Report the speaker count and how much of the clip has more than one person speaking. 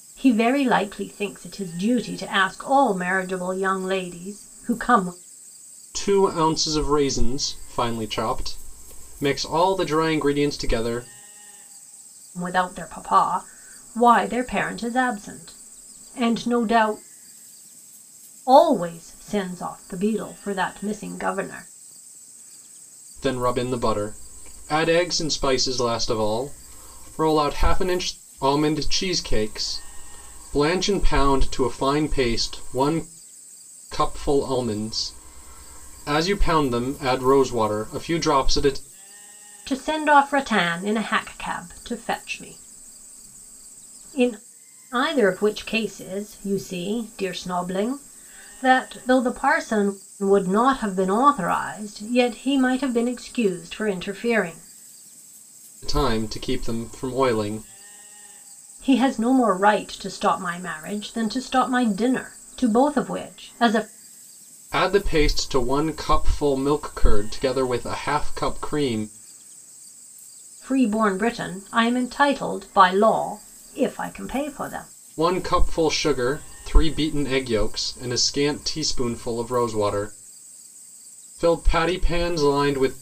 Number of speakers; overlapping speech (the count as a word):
two, no overlap